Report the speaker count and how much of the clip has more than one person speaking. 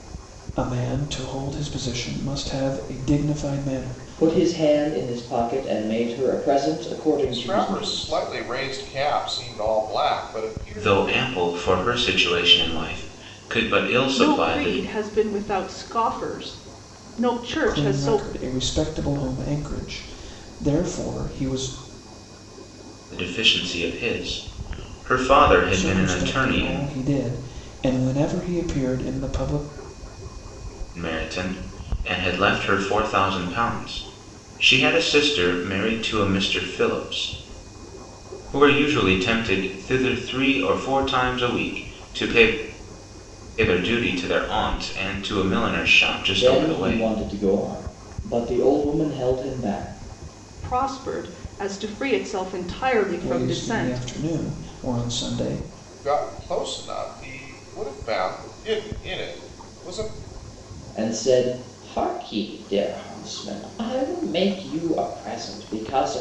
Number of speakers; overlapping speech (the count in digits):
5, about 9%